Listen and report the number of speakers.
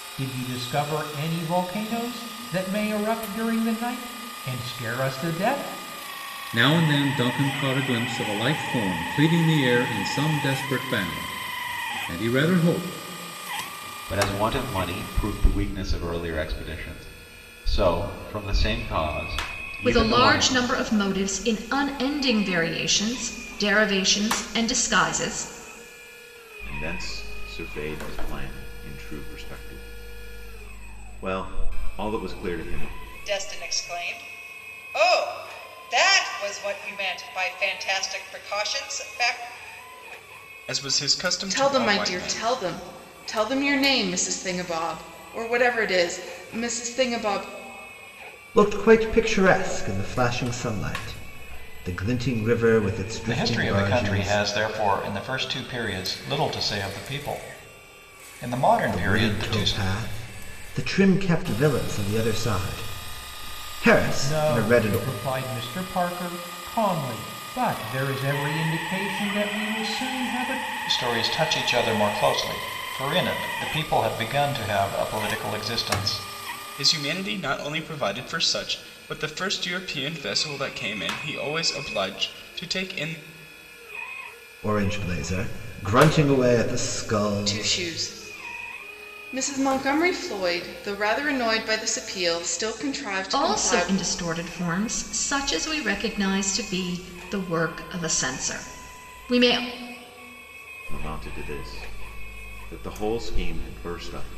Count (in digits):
10